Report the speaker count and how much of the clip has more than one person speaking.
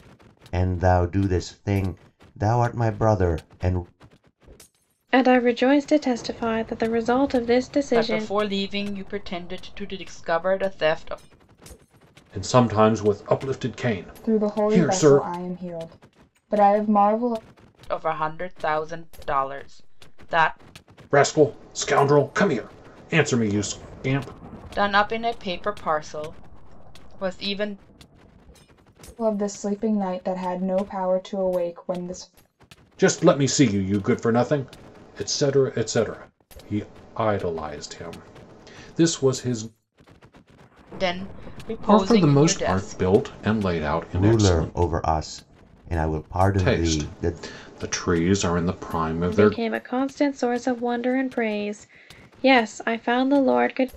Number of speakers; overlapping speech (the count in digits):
5, about 9%